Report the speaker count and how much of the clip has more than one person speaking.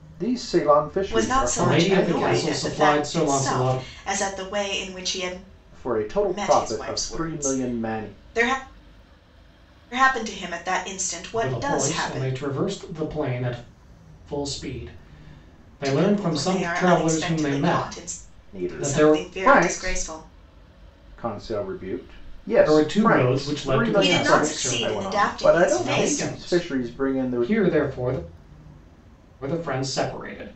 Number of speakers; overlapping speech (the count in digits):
3, about 47%